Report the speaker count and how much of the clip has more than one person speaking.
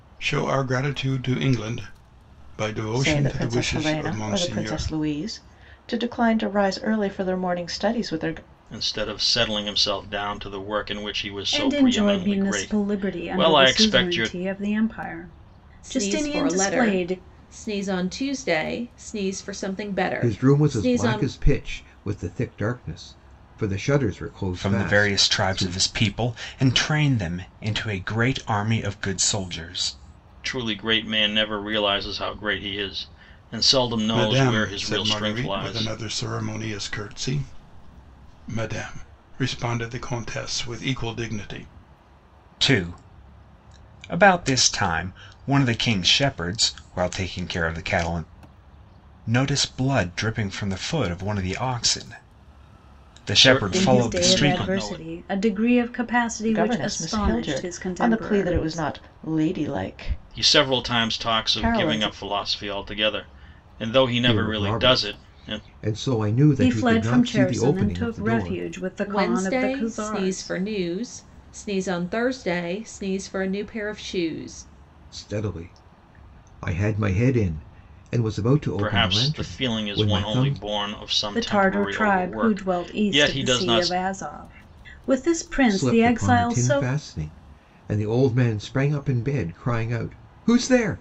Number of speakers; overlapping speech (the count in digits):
7, about 30%